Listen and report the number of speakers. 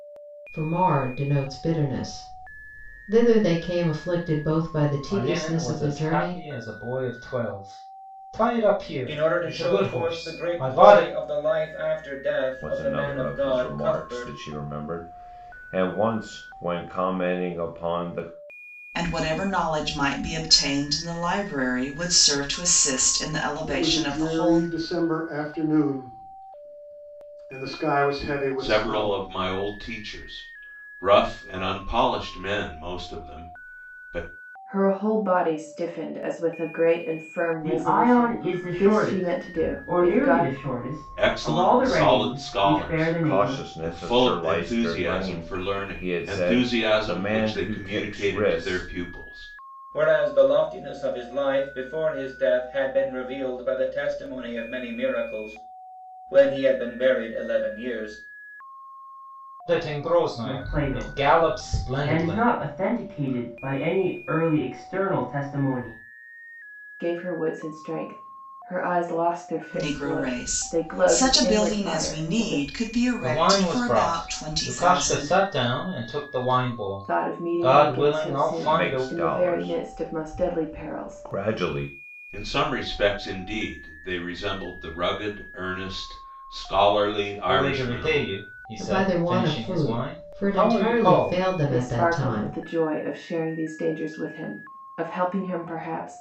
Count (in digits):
9